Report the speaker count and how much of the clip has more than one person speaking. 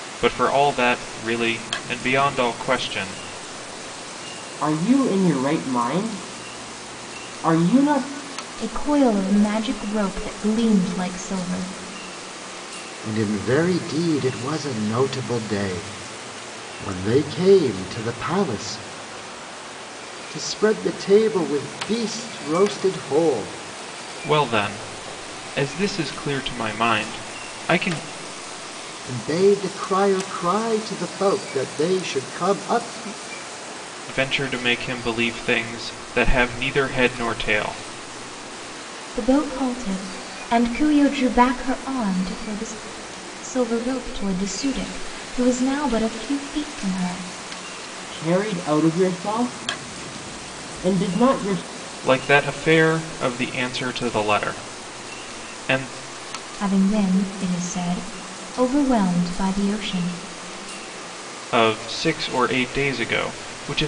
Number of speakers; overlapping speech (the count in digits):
4, no overlap